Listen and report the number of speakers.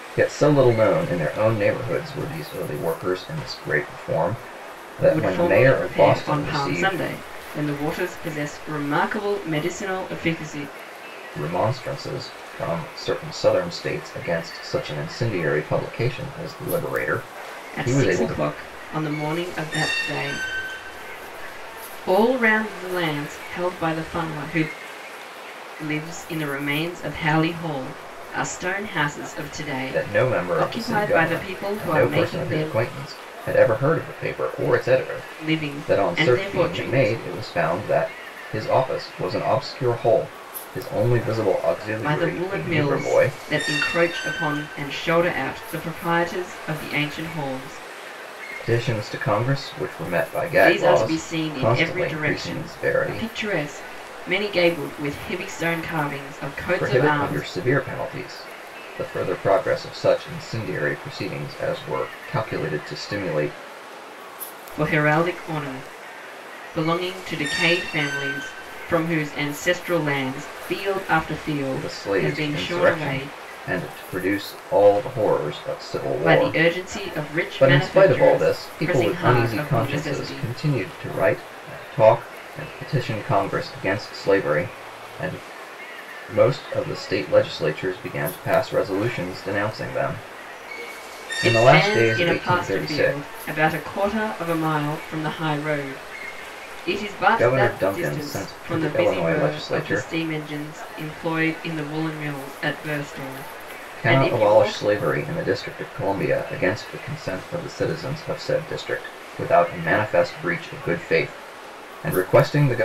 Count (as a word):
two